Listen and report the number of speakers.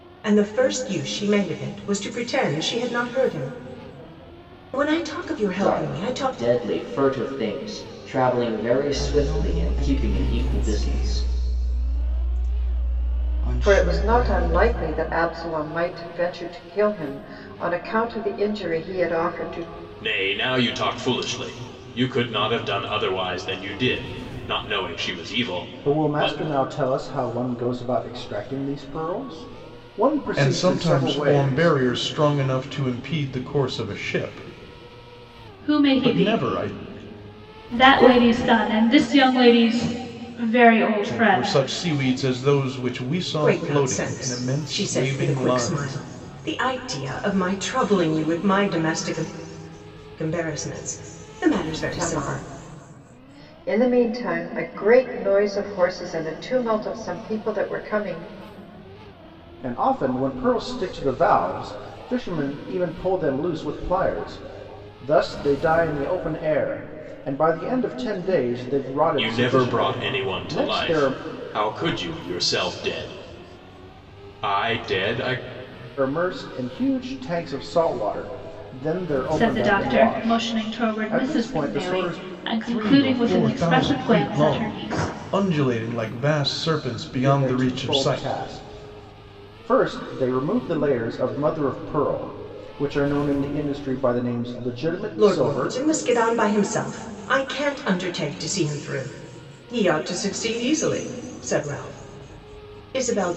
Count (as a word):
eight